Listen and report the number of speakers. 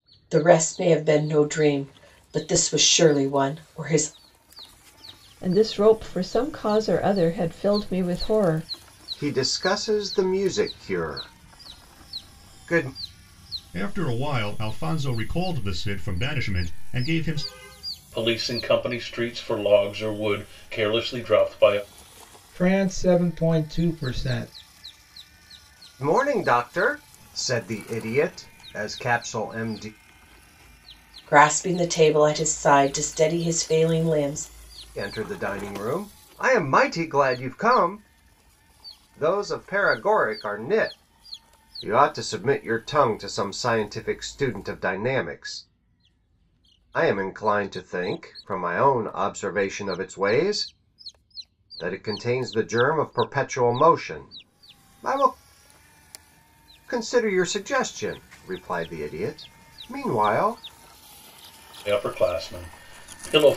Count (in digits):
6